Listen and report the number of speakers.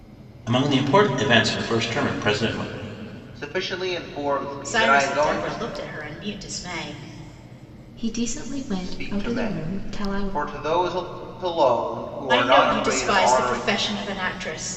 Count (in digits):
4